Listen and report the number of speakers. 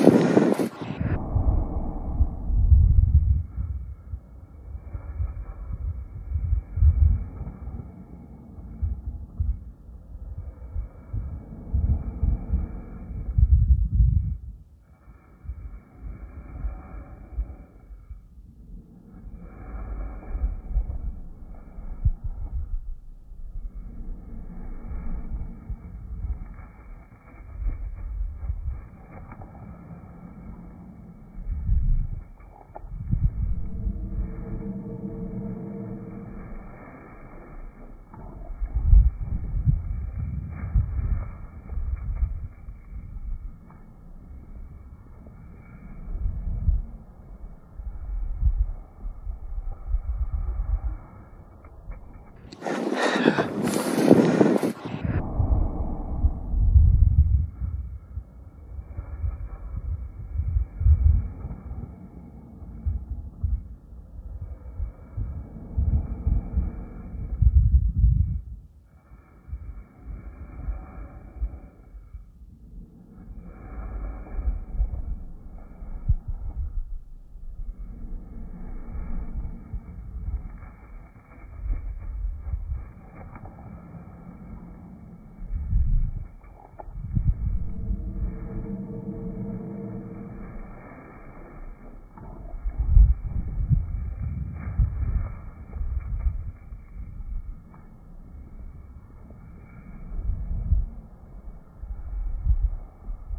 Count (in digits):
0